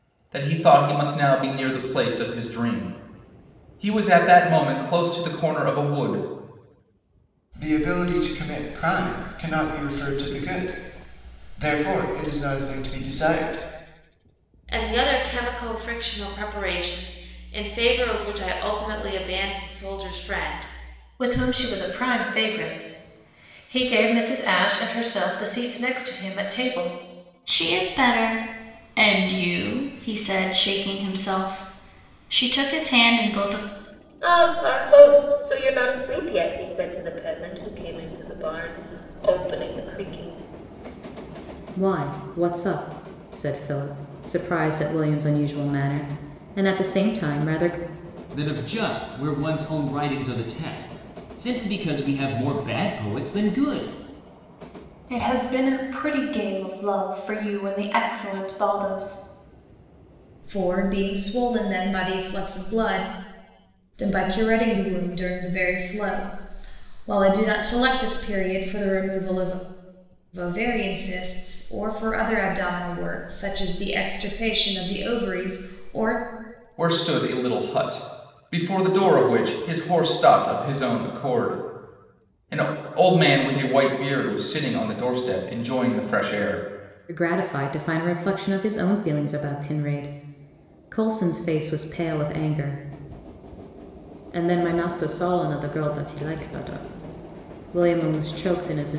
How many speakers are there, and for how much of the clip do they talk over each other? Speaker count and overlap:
ten, no overlap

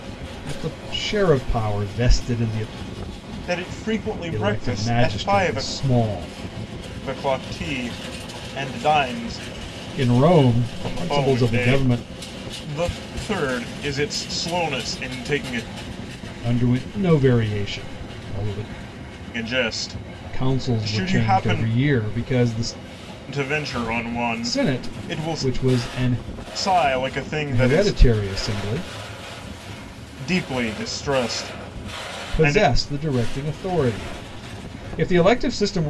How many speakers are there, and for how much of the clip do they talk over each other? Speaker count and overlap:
two, about 16%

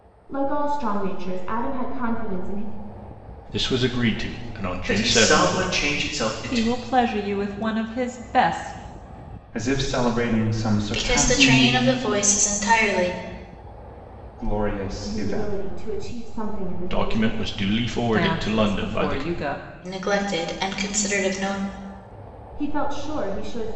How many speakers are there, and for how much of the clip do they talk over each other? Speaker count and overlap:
six, about 19%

